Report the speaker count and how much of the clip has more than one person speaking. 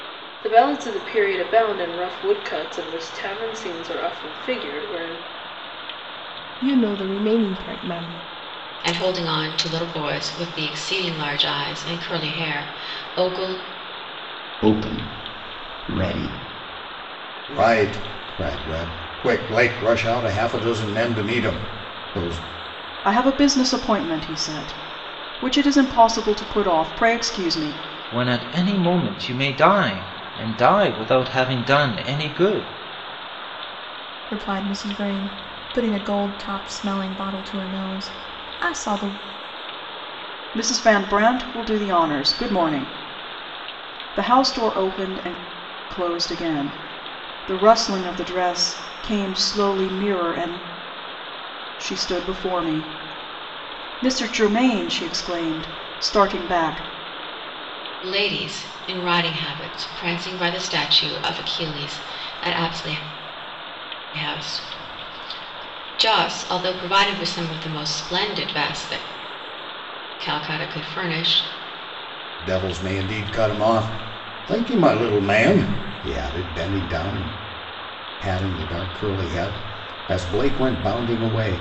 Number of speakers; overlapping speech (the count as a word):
eight, no overlap